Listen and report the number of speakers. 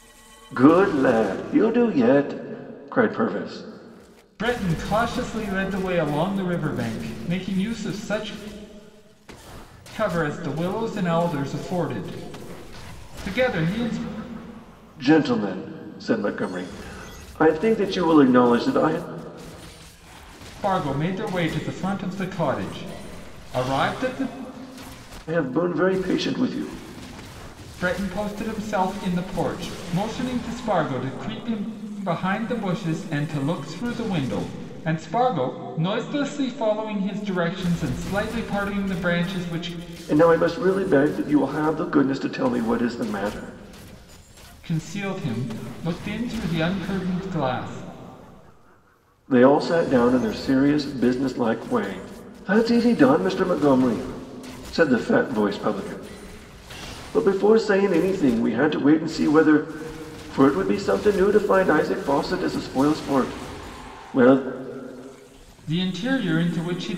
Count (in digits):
2